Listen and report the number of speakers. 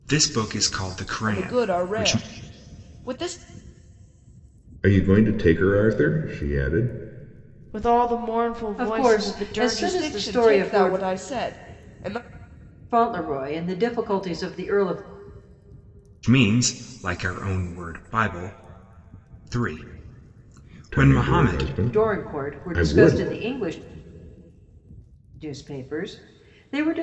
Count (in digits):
5